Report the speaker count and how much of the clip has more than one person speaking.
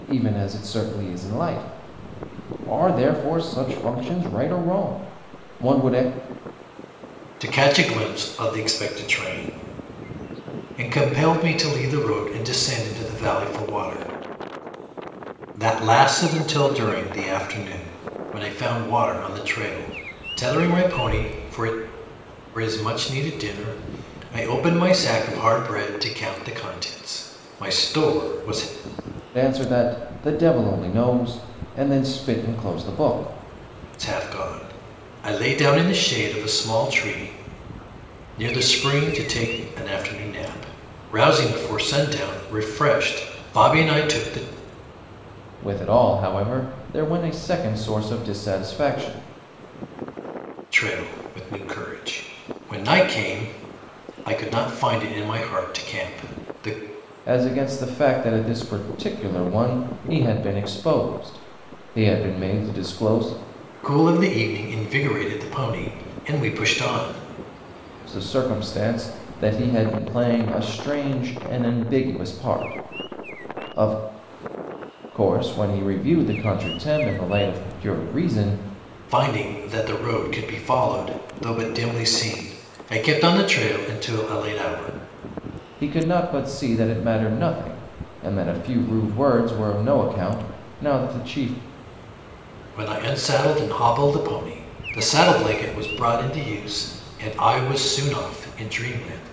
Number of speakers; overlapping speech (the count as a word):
two, no overlap